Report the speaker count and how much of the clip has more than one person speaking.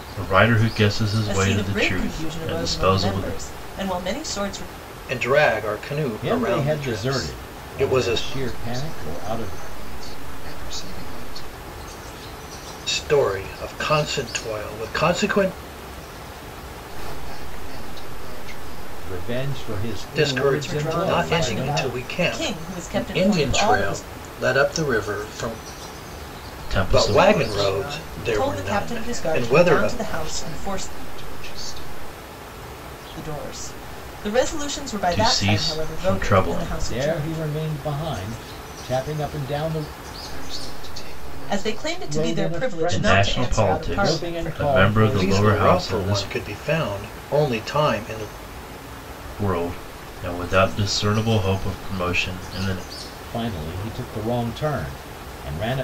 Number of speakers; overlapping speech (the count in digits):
5, about 39%